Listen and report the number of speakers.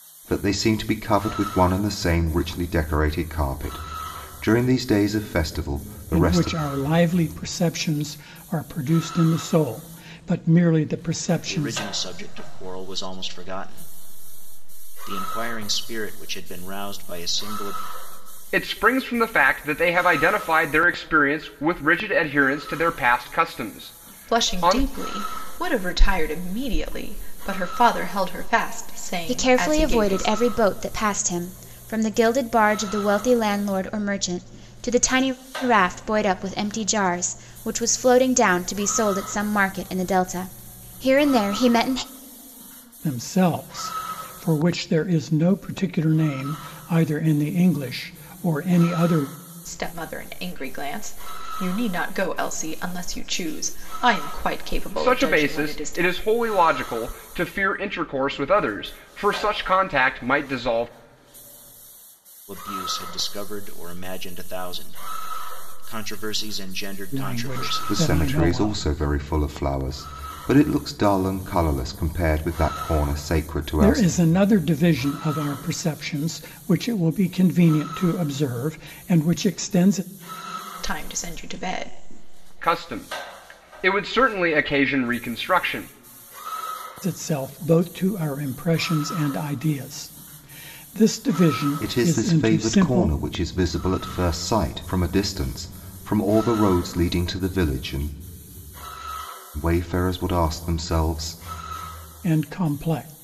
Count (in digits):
6